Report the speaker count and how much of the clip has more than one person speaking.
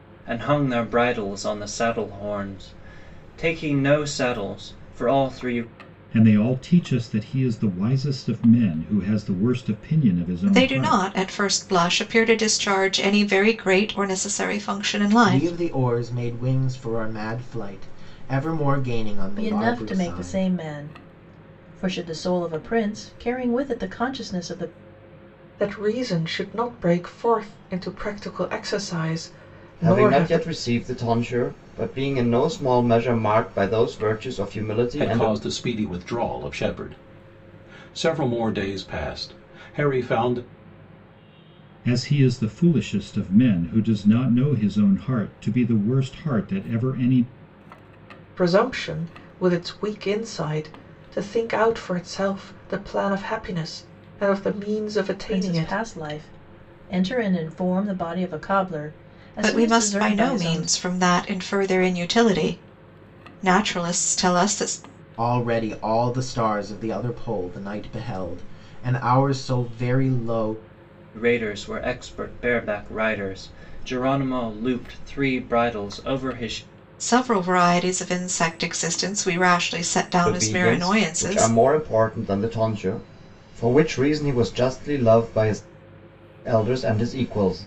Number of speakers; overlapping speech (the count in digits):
8, about 8%